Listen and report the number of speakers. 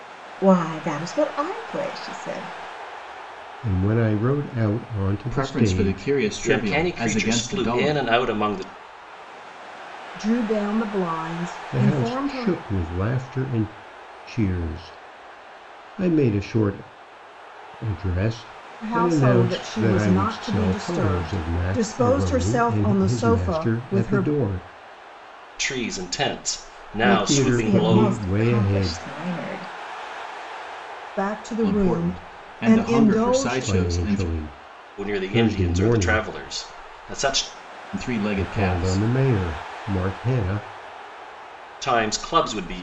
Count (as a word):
five